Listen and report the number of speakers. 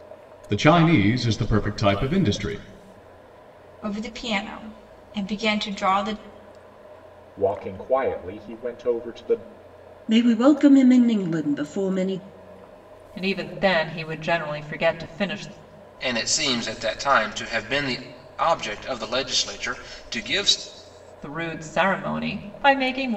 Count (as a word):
six